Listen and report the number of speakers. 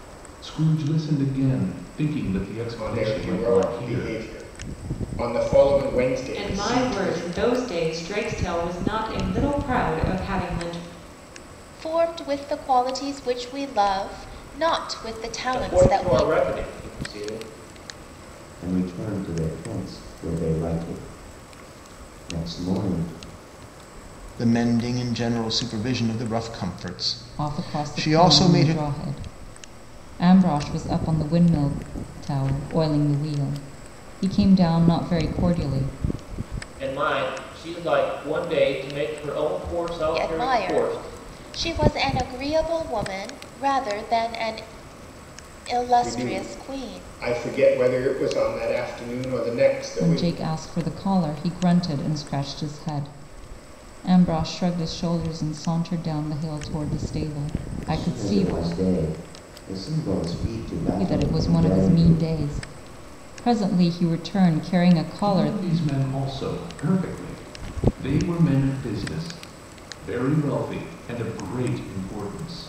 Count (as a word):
eight